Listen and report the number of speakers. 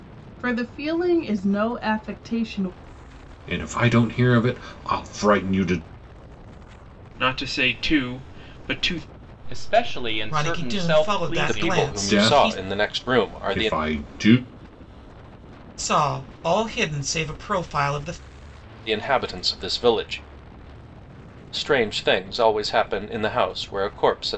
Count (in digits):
6